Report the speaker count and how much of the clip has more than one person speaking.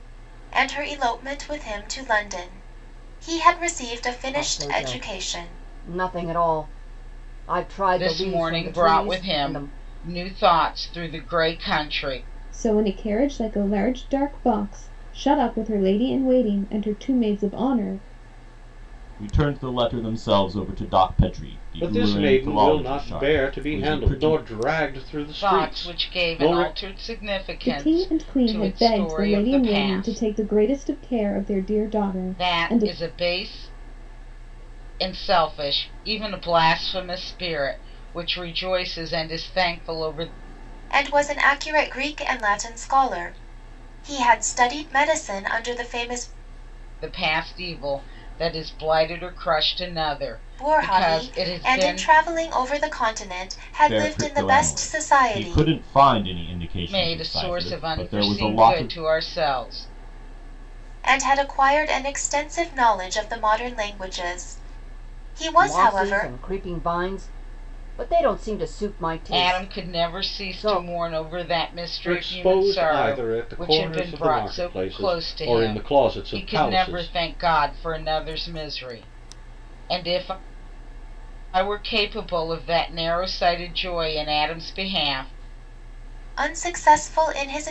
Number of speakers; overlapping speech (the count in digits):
6, about 26%